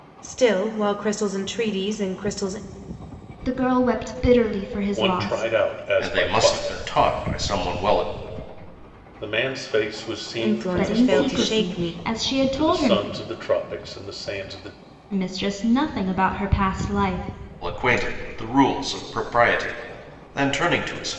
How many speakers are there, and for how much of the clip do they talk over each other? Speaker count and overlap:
4, about 17%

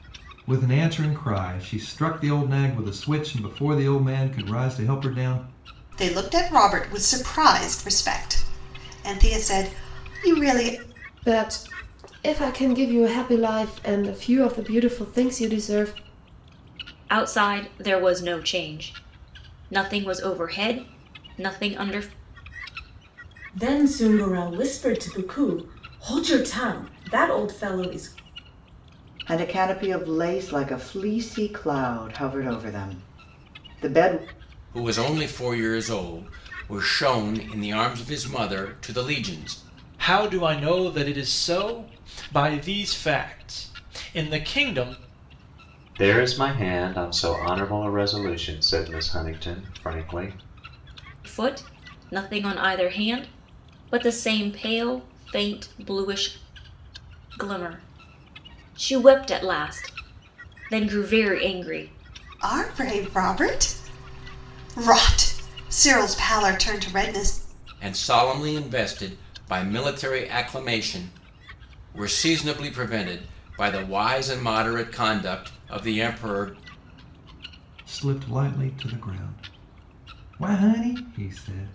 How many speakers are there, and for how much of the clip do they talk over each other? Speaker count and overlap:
9, no overlap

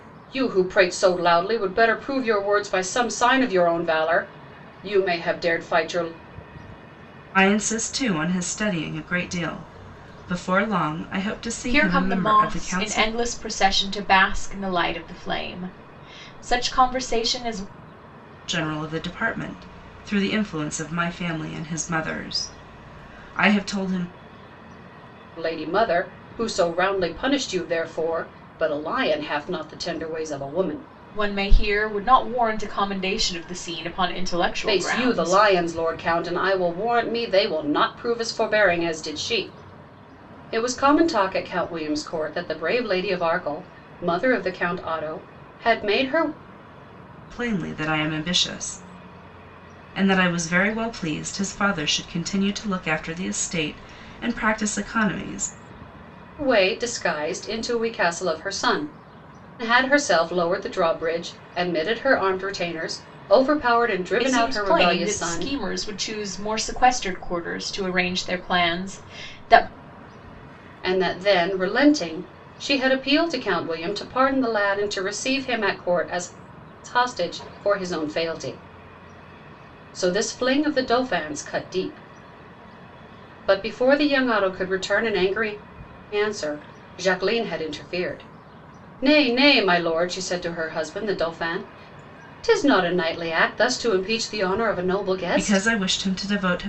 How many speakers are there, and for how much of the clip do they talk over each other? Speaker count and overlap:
3, about 4%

